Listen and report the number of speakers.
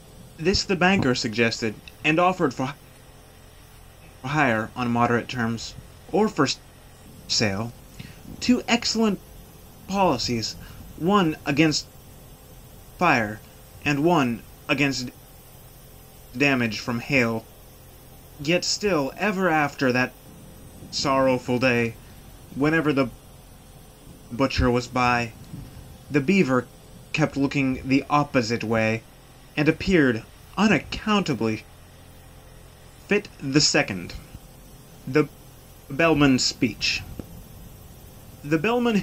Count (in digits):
1